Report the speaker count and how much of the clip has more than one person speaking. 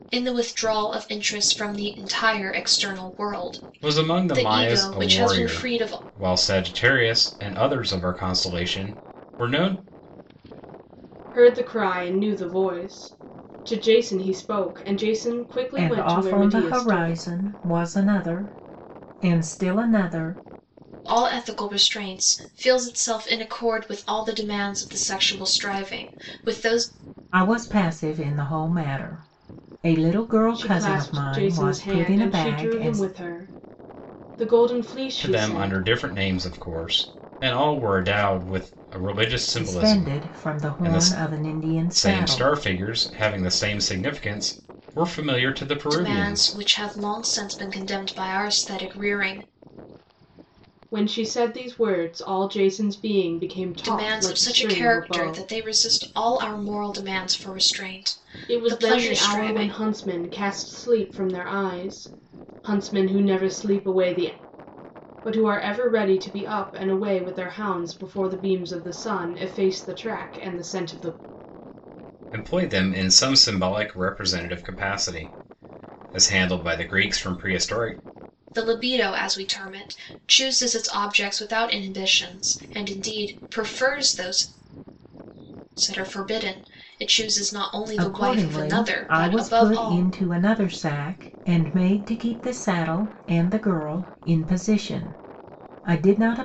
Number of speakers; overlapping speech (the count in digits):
4, about 16%